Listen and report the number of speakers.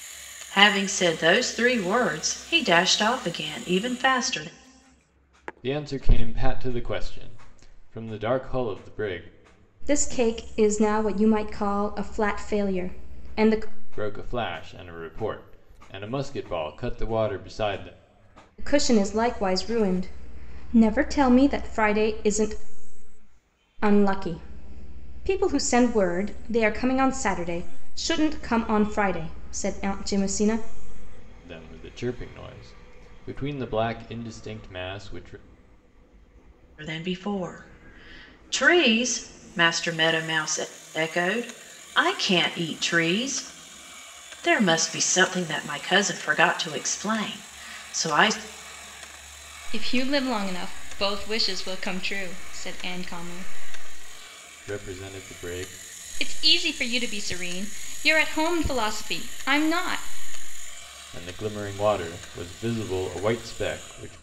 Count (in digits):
3